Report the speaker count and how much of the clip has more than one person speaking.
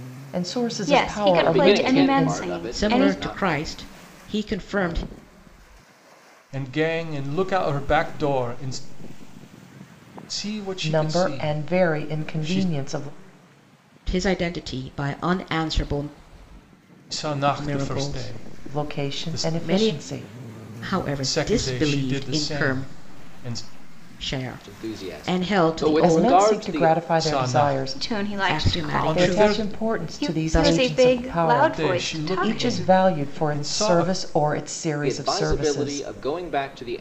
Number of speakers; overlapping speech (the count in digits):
5, about 51%